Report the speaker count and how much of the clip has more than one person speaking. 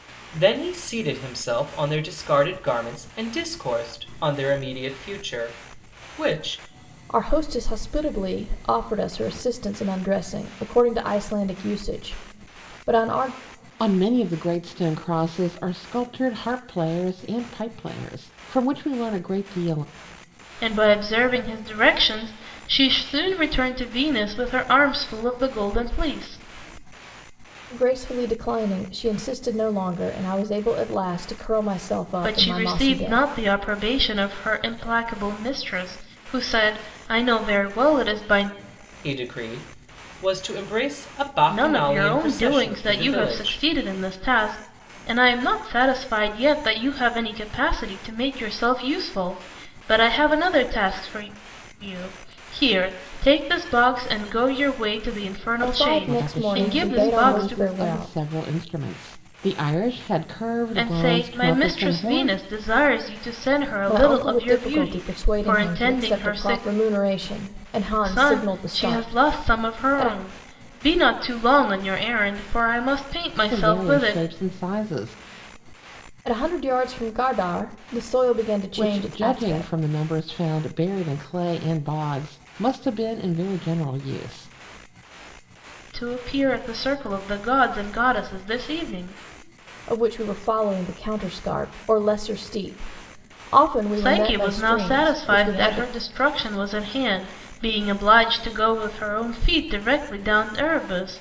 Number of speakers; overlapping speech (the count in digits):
4, about 16%